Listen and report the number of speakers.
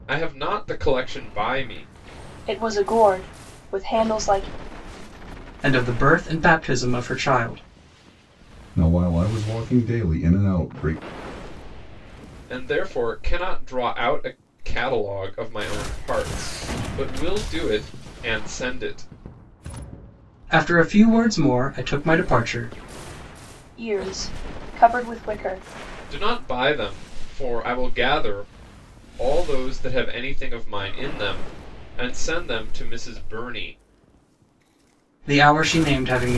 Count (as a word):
four